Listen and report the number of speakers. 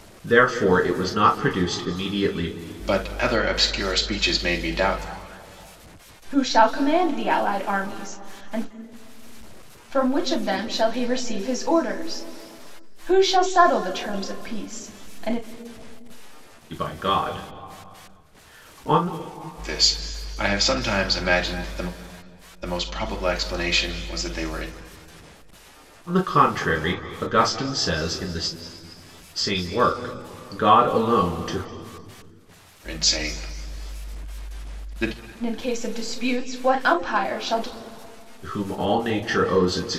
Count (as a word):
three